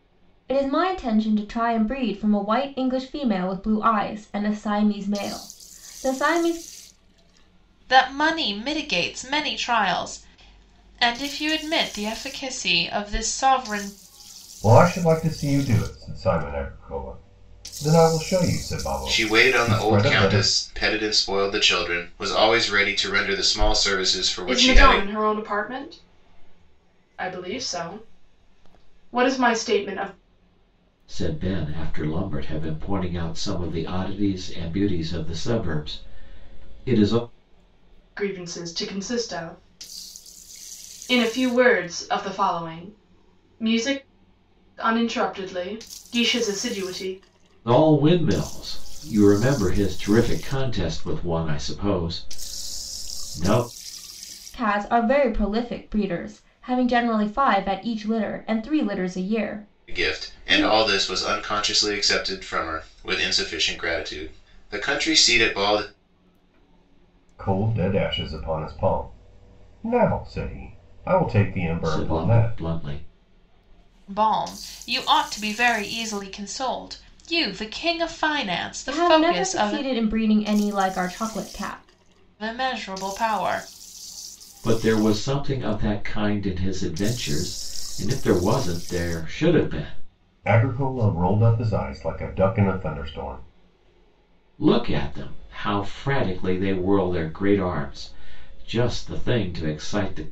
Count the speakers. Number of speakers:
six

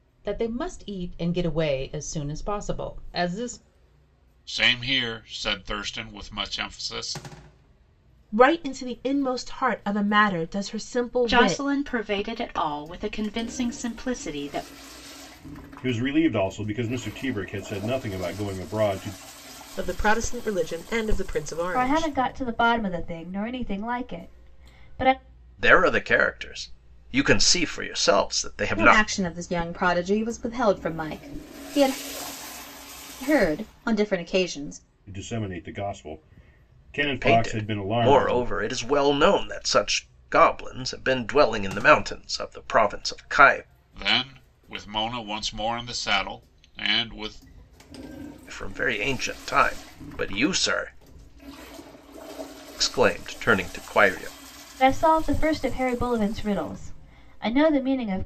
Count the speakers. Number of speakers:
nine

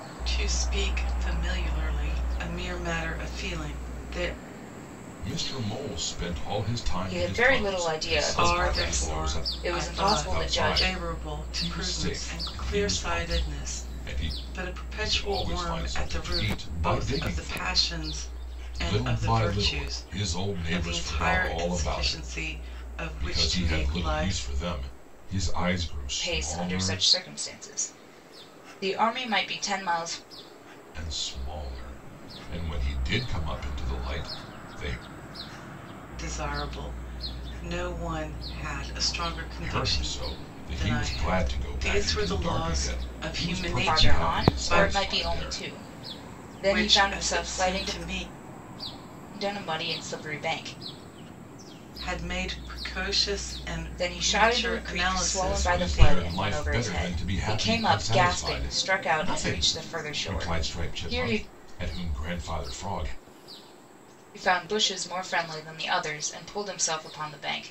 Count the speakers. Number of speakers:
three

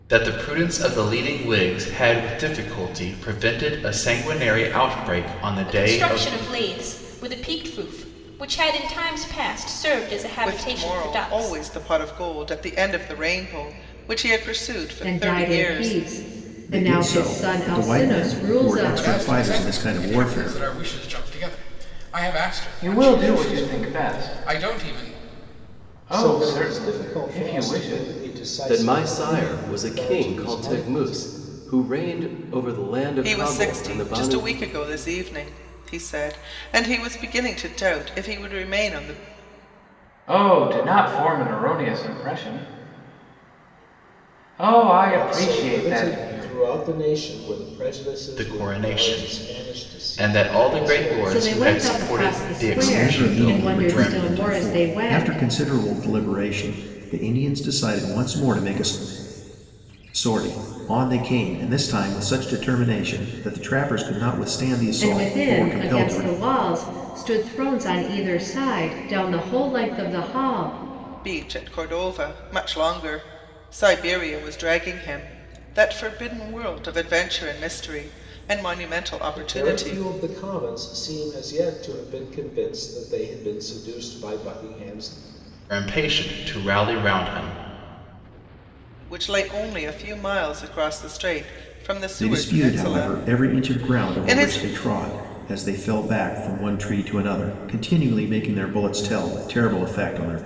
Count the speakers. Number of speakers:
nine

